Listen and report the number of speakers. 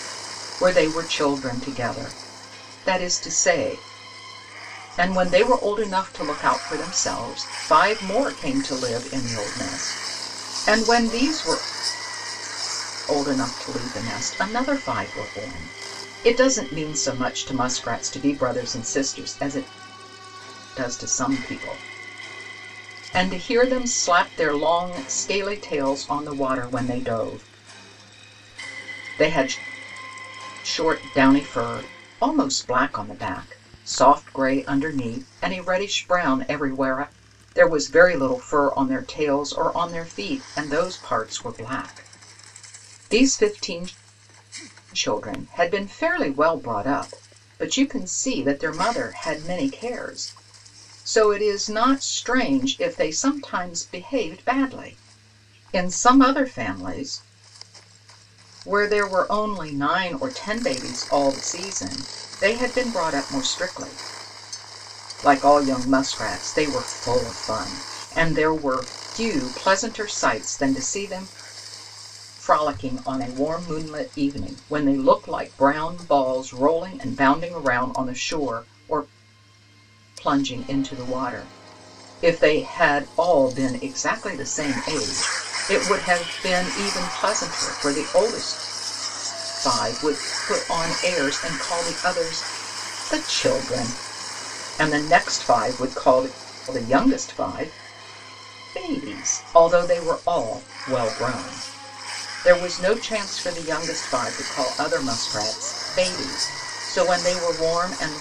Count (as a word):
one